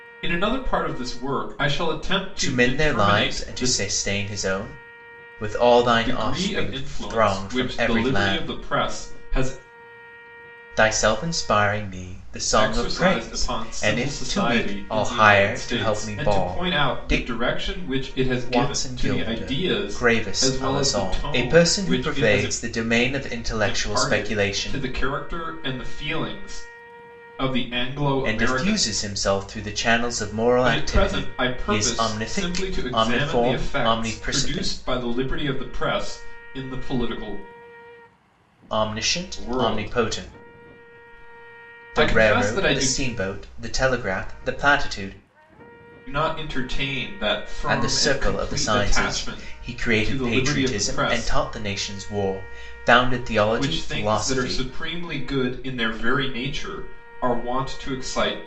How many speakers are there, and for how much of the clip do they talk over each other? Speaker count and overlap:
2, about 43%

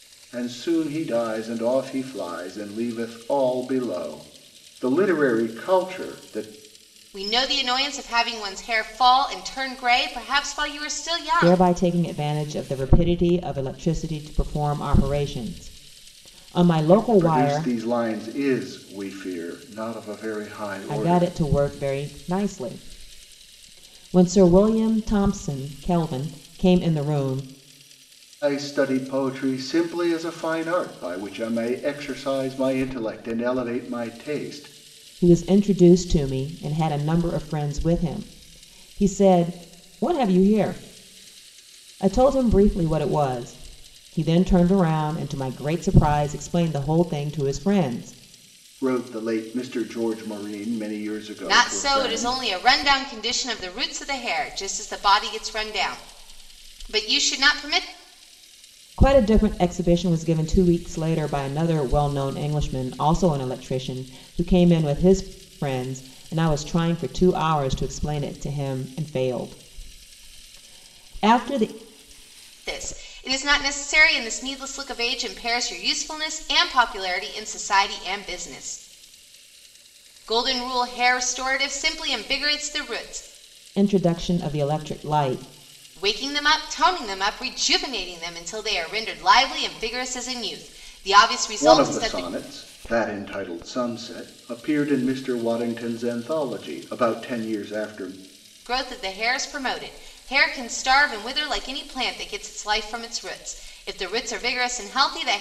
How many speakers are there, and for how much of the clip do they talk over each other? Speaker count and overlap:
3, about 3%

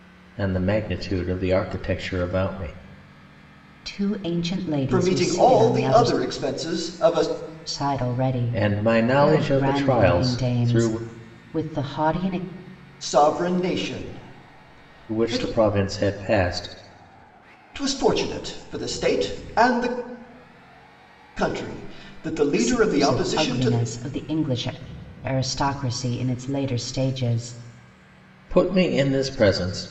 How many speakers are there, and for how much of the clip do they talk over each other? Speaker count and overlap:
3, about 18%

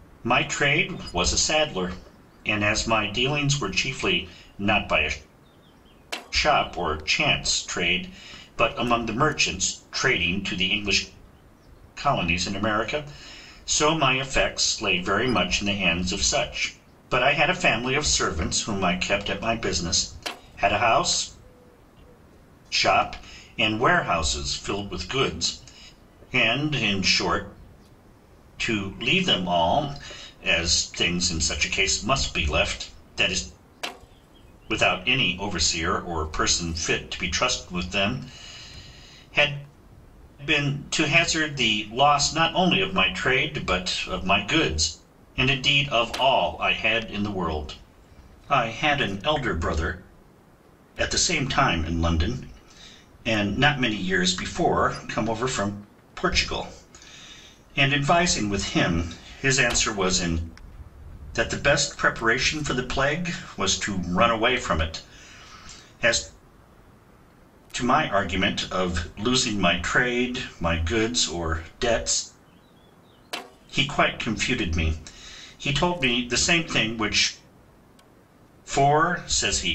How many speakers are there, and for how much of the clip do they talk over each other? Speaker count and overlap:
1, no overlap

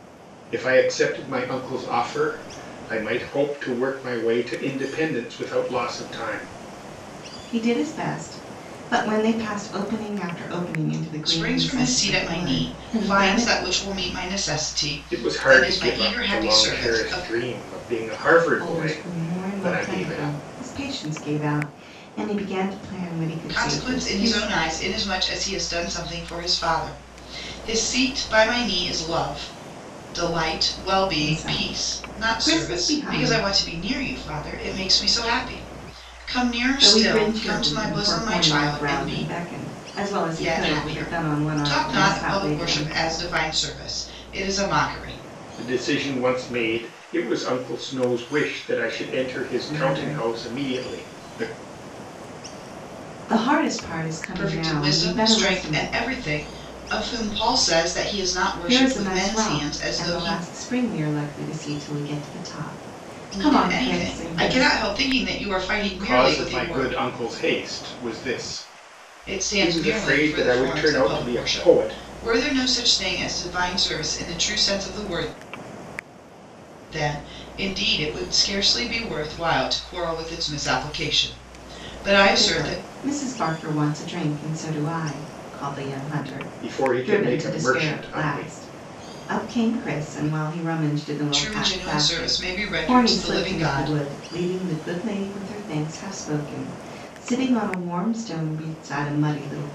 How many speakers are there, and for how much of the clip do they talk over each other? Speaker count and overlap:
3, about 31%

